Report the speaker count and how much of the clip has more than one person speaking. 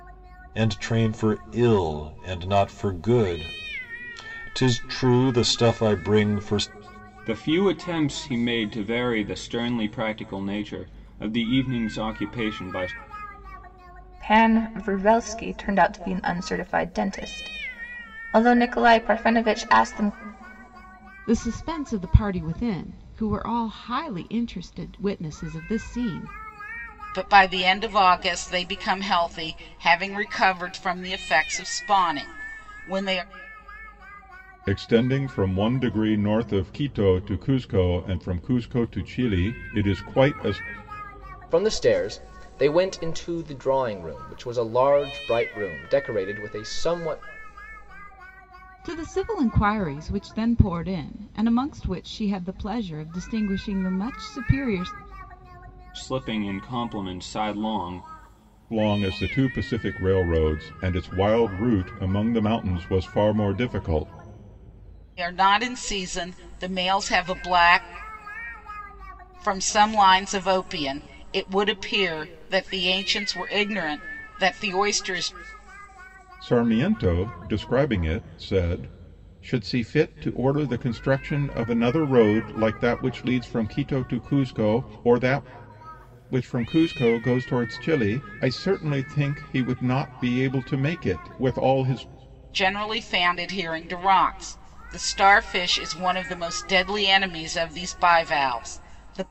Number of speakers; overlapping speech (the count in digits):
7, no overlap